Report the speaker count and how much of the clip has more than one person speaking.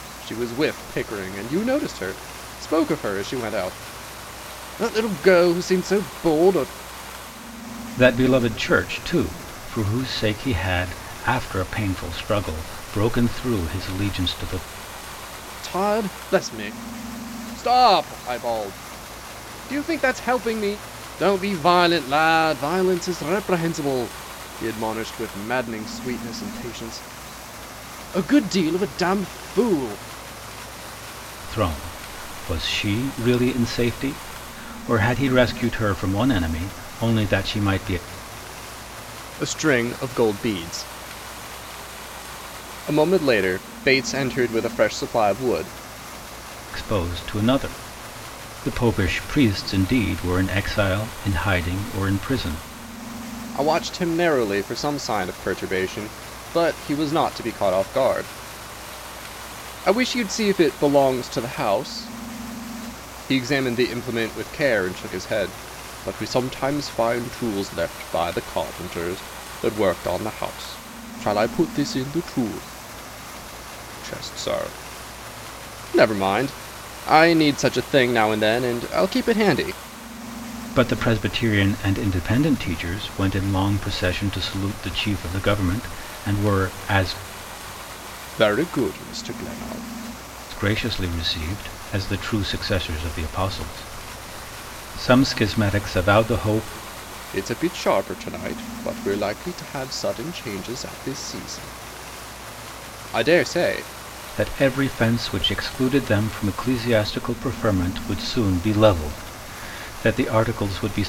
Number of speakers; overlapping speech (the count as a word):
two, no overlap